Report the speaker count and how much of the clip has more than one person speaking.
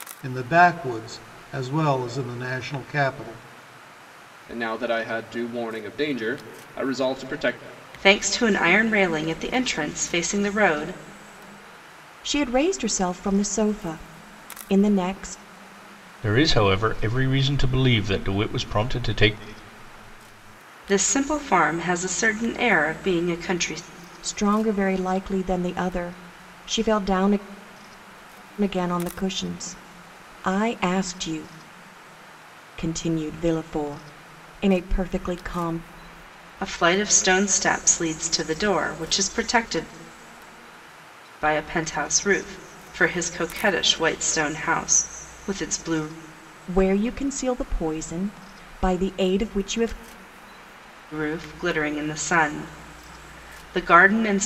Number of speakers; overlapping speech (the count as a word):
five, no overlap